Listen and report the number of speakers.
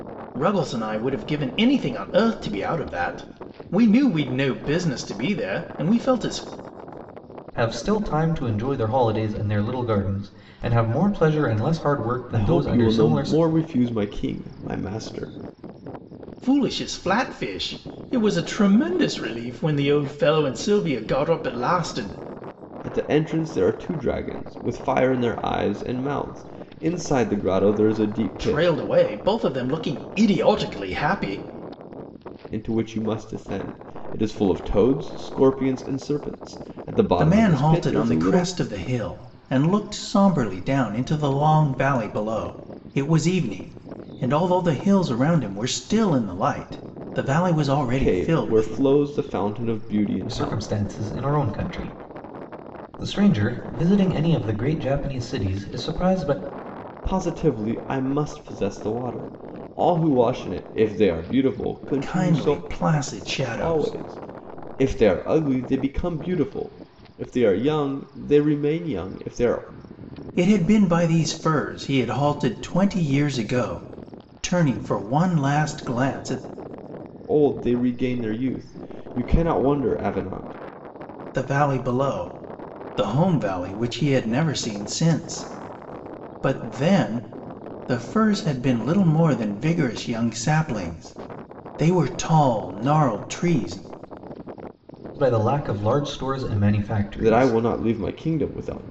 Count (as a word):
three